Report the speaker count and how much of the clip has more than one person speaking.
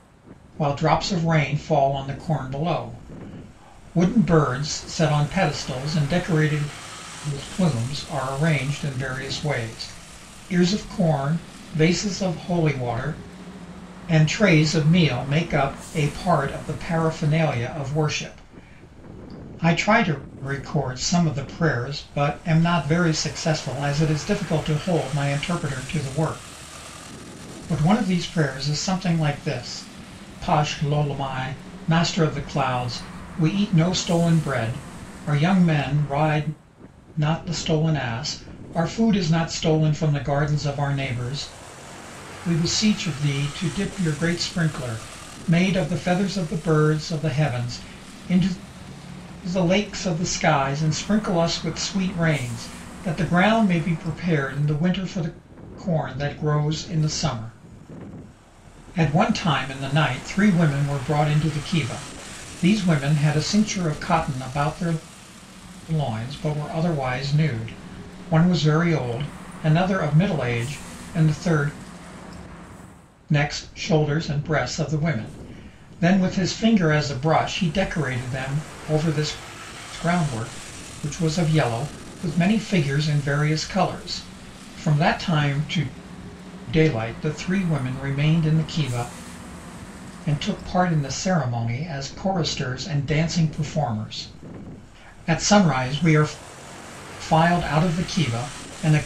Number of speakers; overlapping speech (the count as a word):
one, no overlap